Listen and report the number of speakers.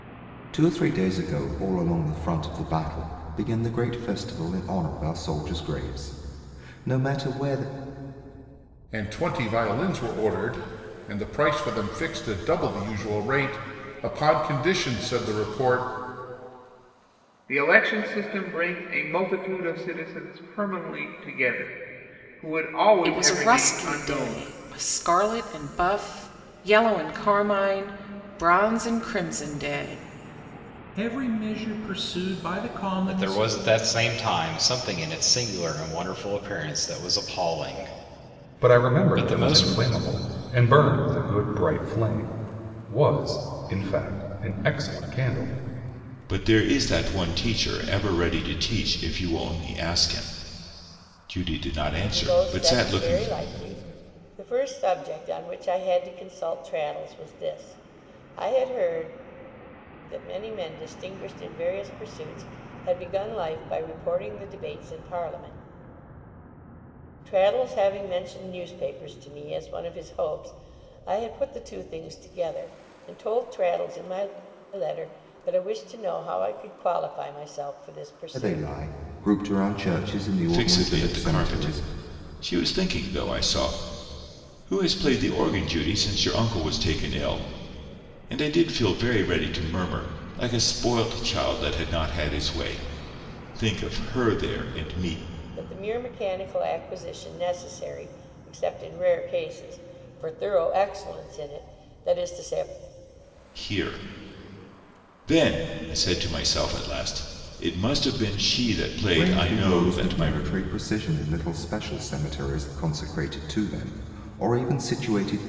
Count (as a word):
nine